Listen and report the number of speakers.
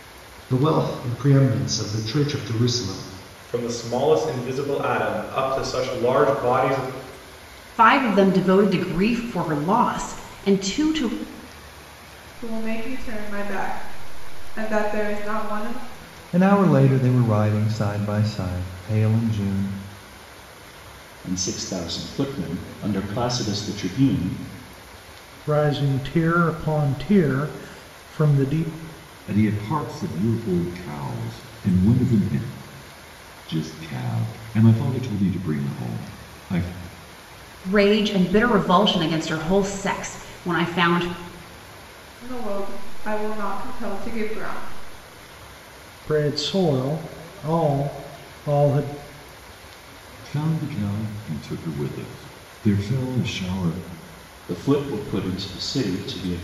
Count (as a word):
eight